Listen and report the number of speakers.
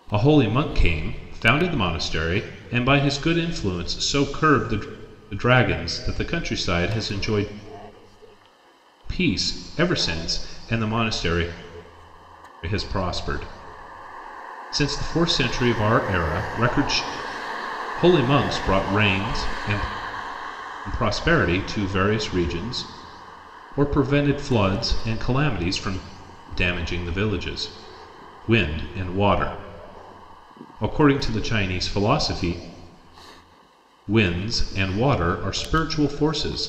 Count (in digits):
1